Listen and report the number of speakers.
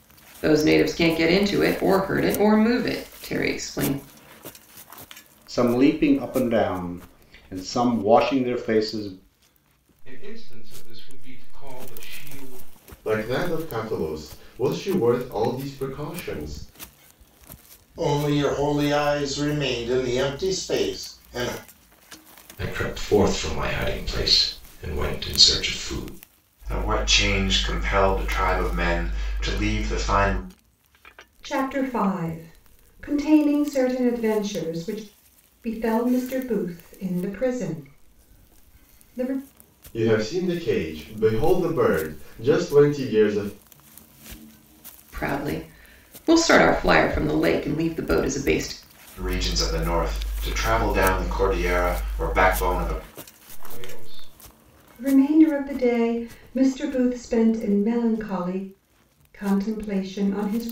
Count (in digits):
8